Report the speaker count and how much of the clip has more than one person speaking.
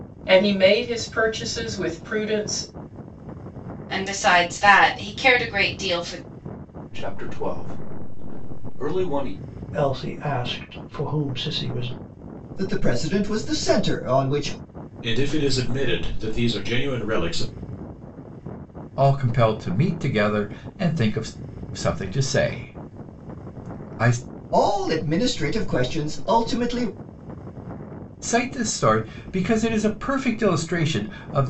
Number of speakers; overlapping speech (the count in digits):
7, no overlap